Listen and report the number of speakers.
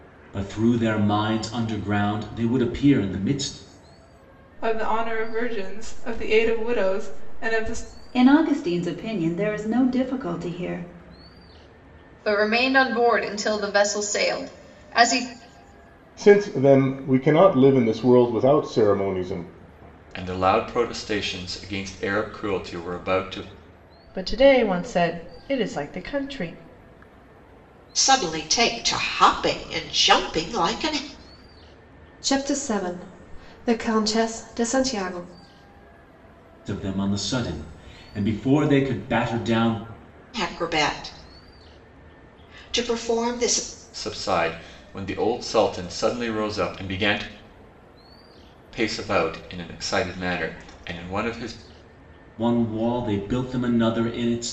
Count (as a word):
nine